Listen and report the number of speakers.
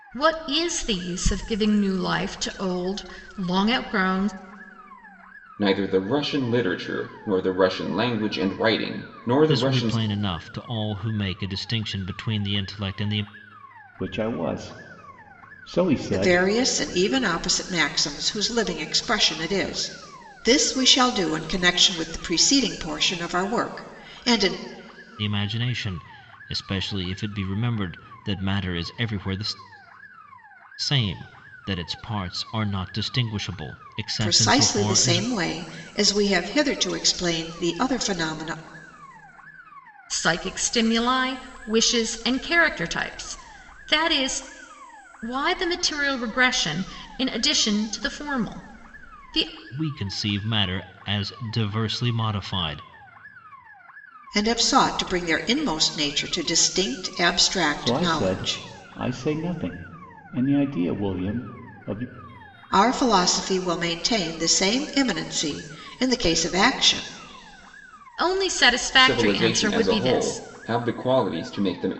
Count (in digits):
5